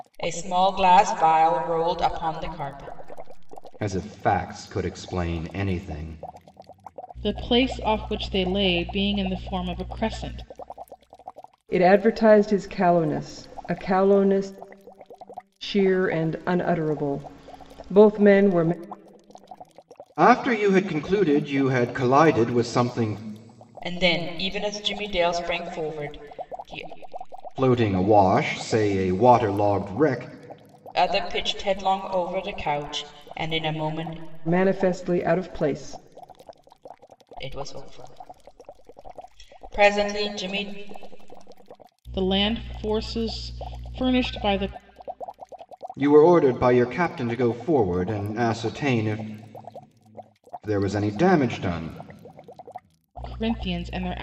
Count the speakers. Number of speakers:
4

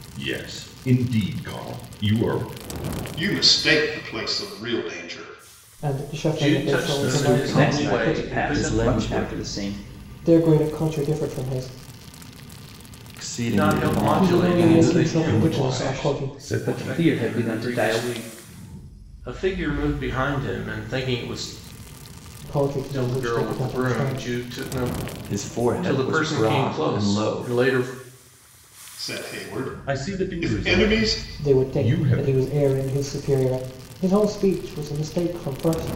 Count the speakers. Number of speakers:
6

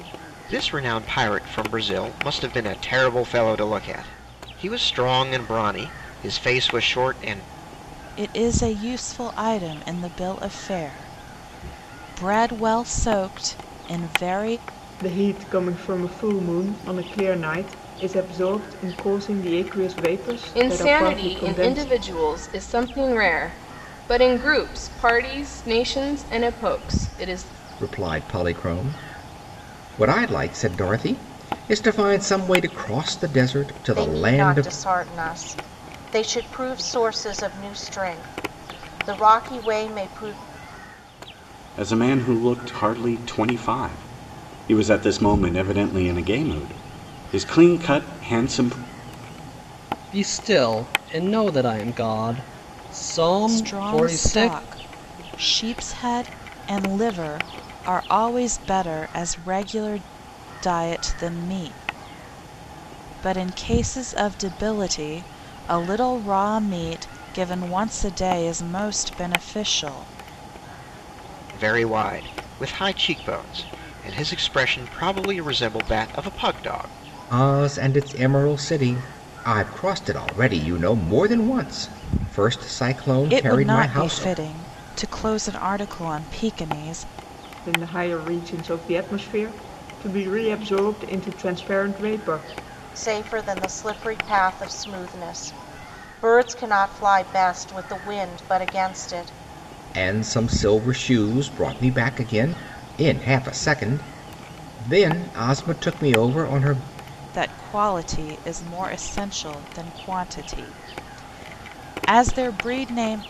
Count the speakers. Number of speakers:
8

